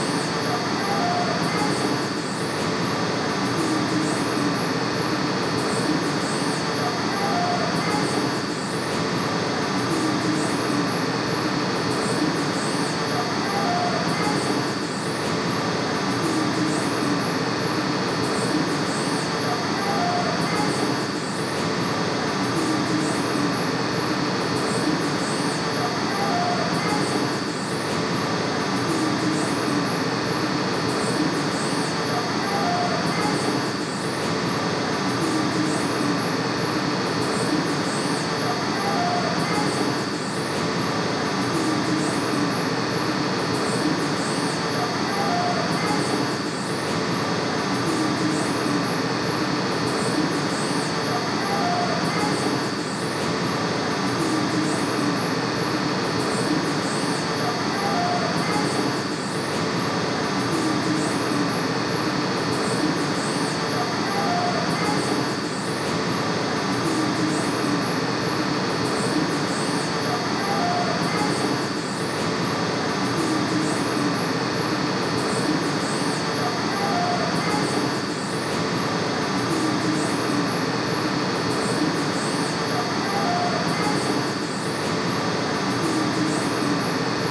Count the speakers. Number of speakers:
0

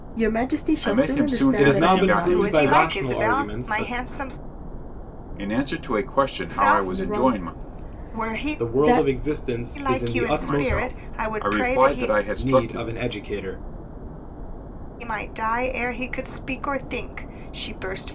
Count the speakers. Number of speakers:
4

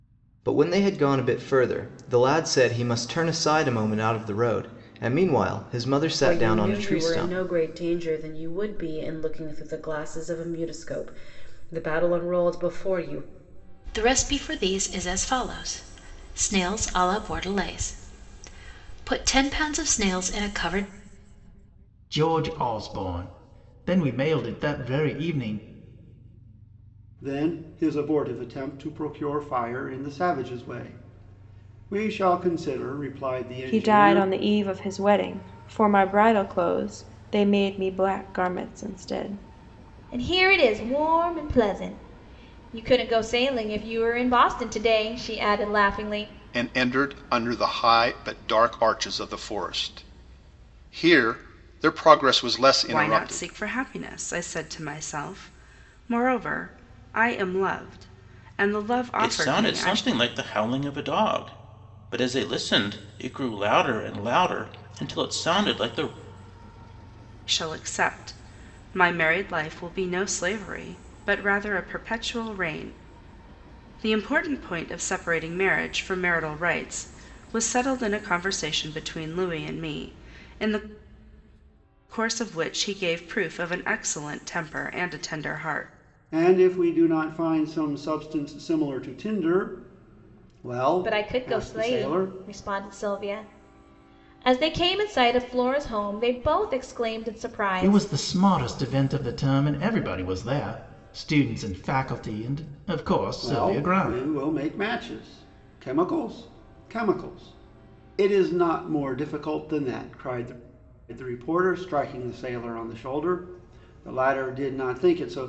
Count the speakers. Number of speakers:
10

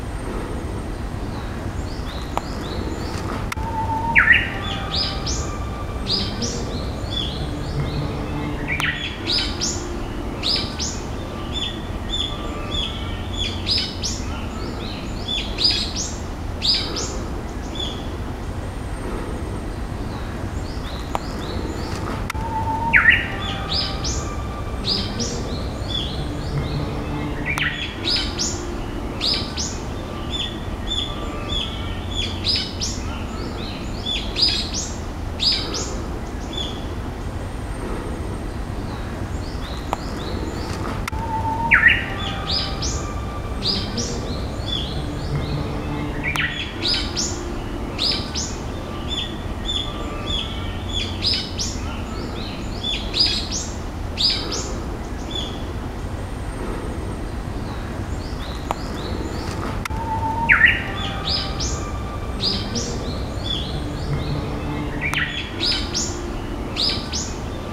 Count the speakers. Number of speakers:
0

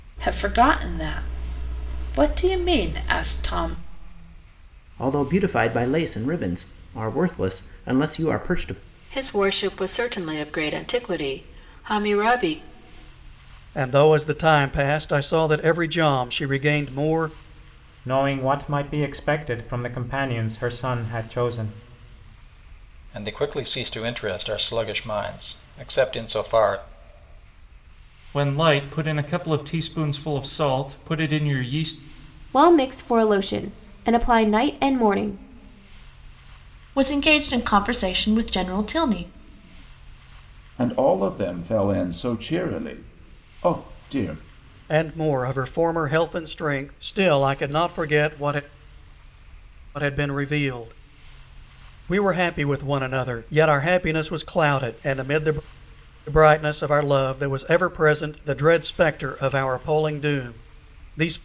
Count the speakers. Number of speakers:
10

